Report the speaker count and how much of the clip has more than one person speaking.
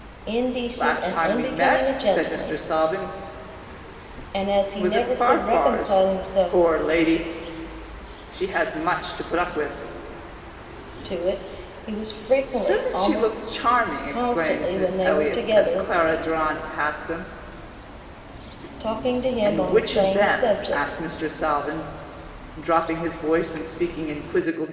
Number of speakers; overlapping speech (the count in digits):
2, about 32%